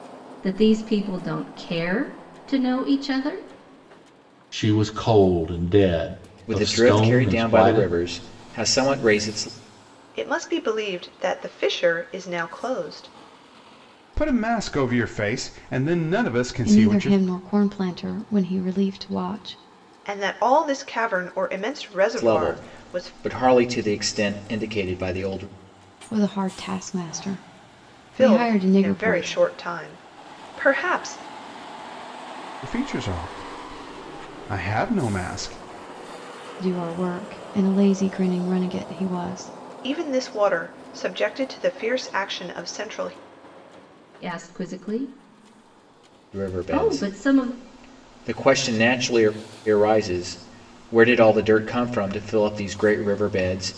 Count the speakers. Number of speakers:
six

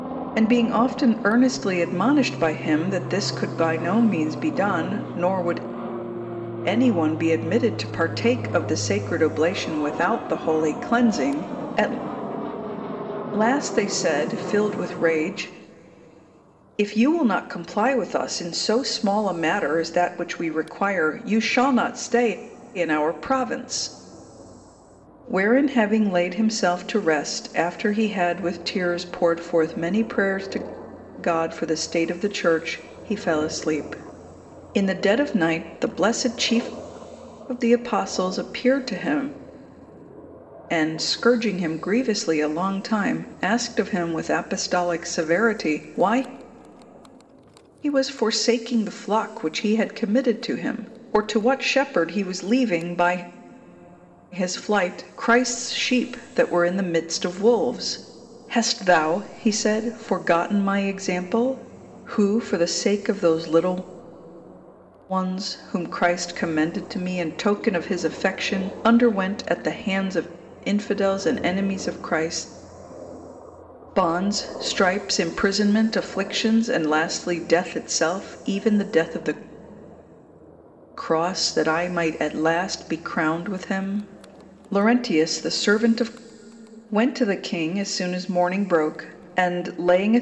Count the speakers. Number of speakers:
one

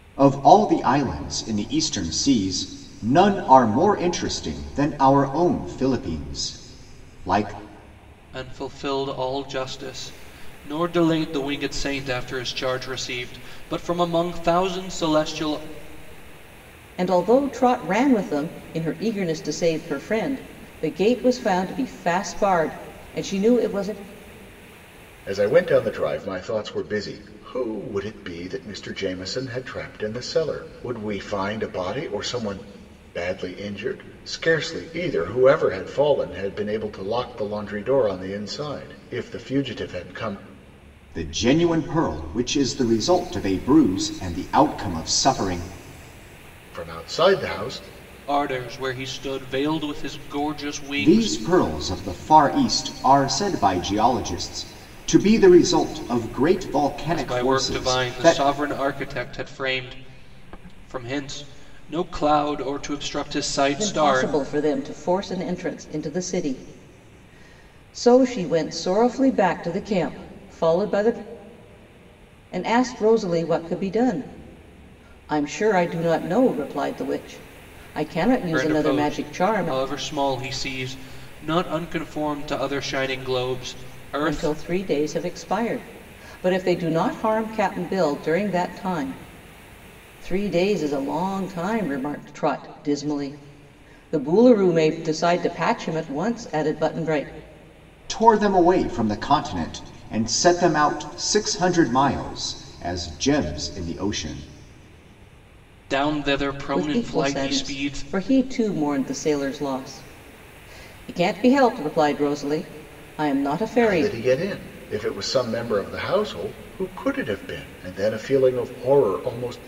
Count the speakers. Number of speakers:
four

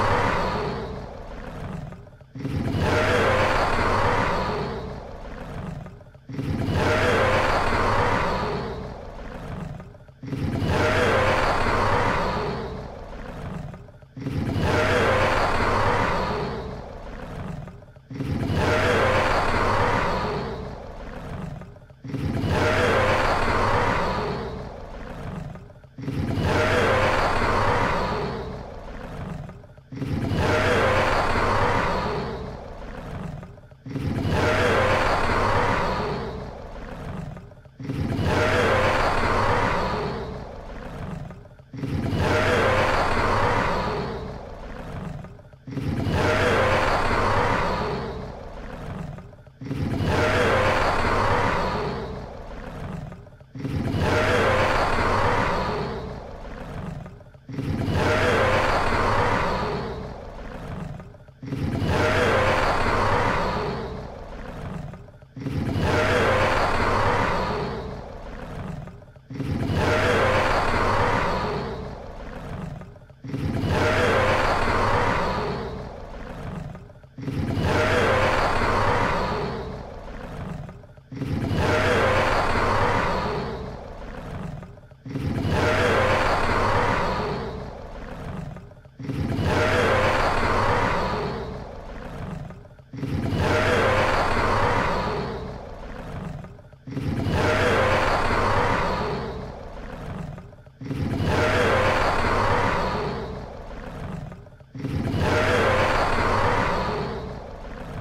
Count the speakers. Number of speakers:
zero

